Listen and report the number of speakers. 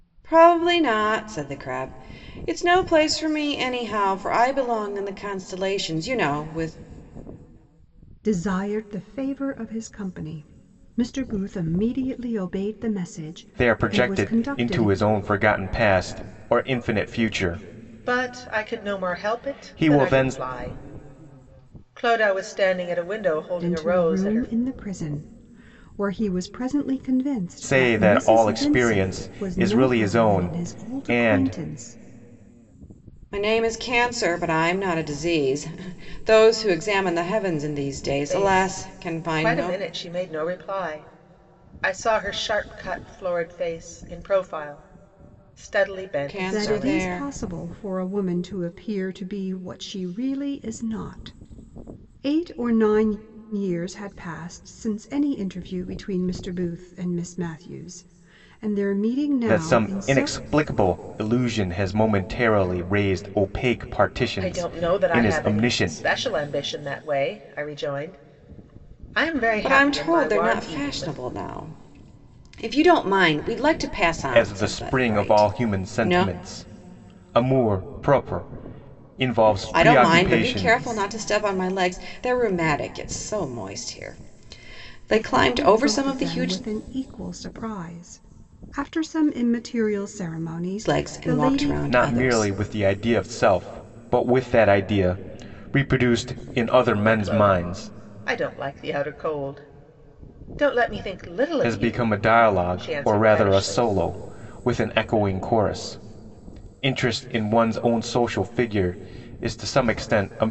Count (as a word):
four